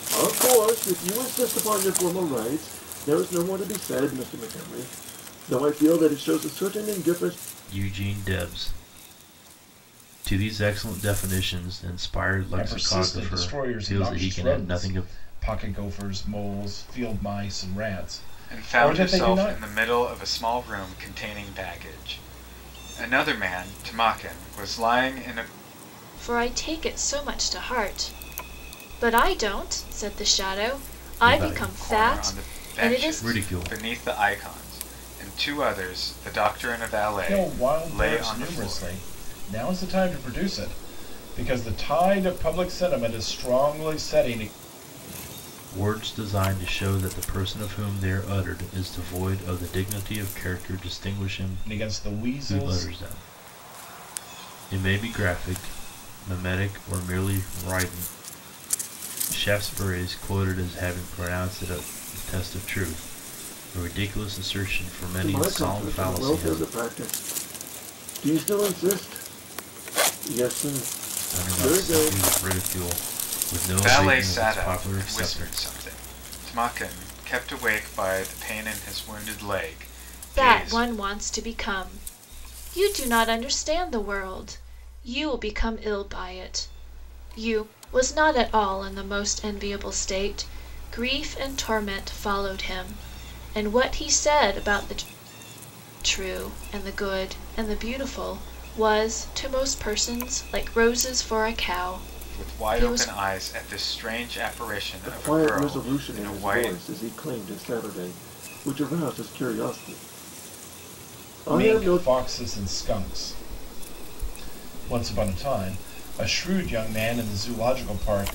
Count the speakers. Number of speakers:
5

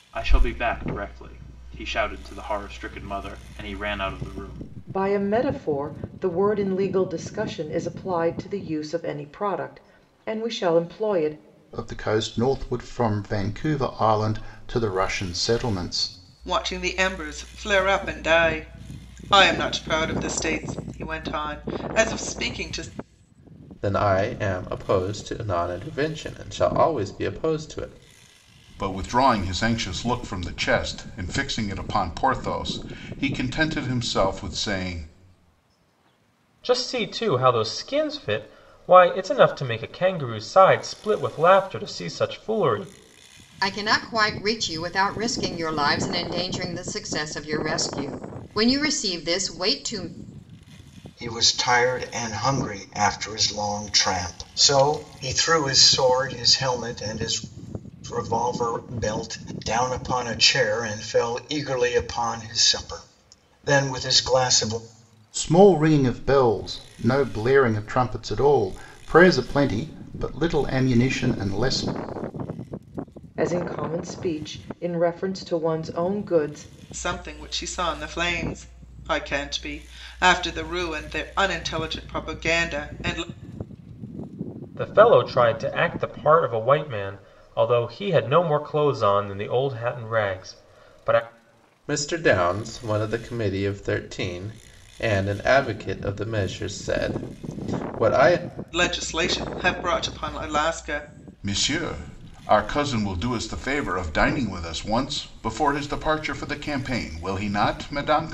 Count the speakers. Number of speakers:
9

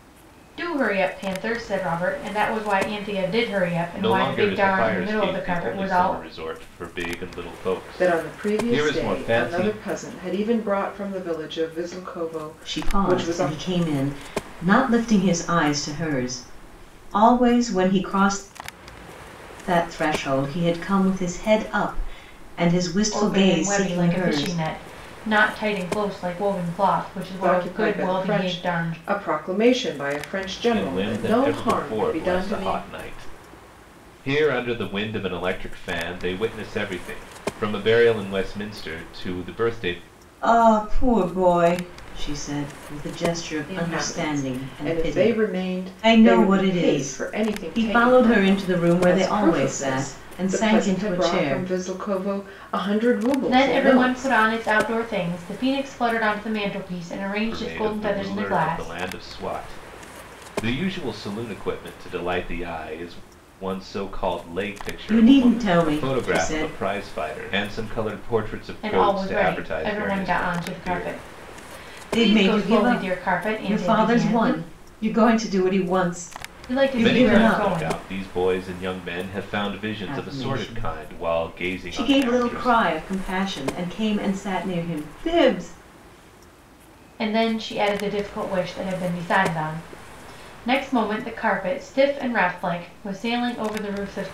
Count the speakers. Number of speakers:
4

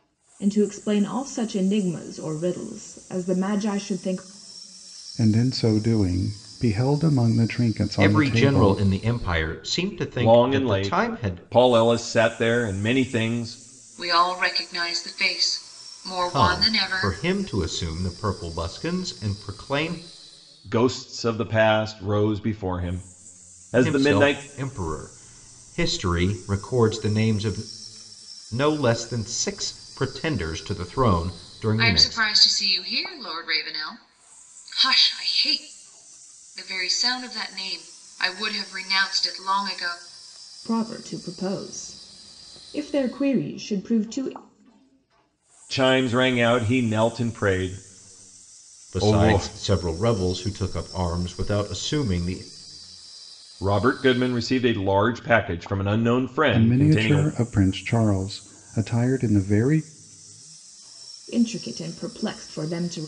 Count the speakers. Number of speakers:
5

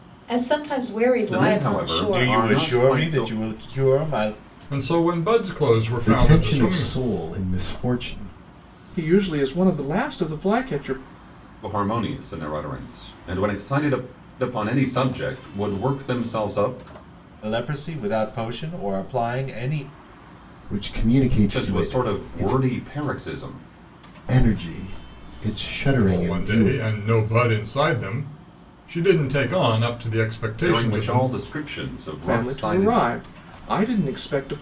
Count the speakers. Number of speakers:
6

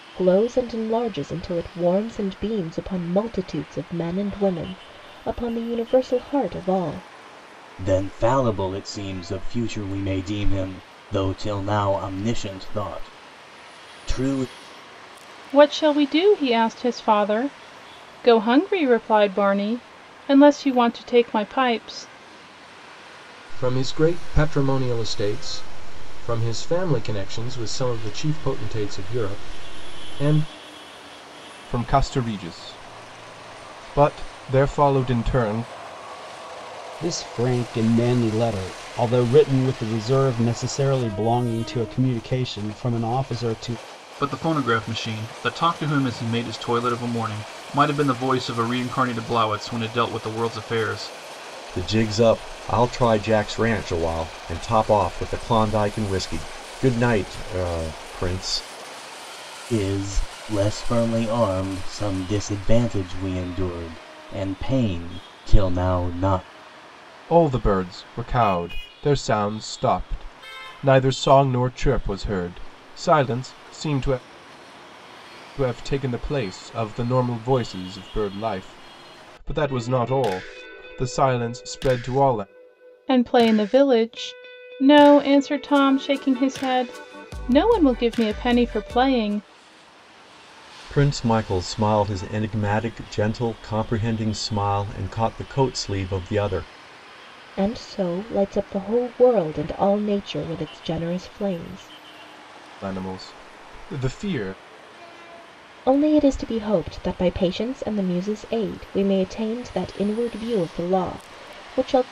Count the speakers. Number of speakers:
8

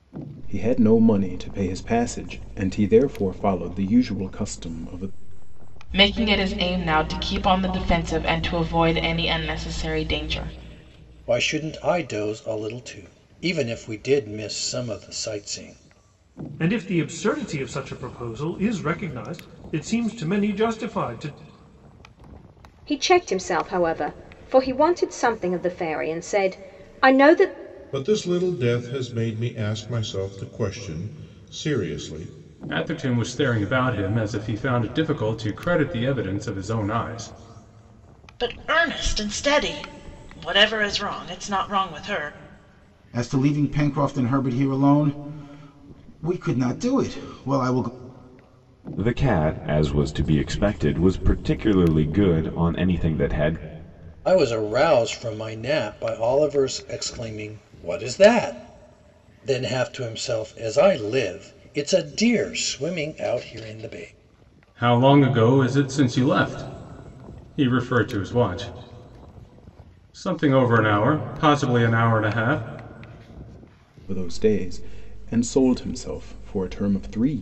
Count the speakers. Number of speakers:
10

